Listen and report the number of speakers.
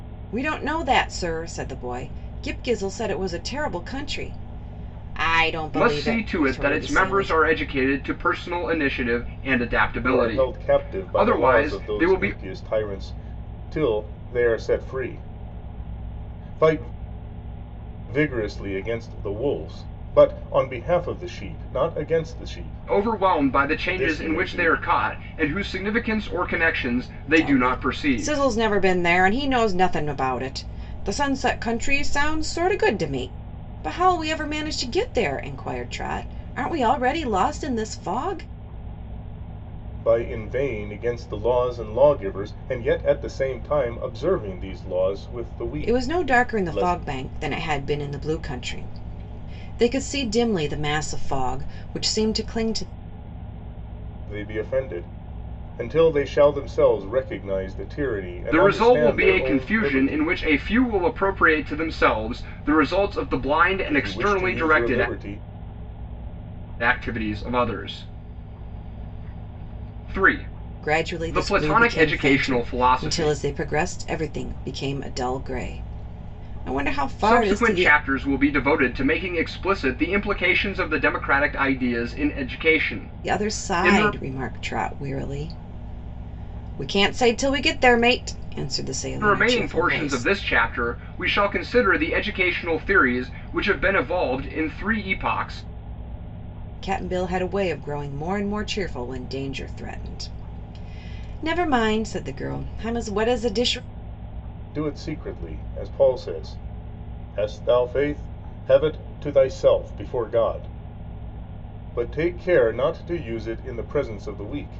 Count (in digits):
3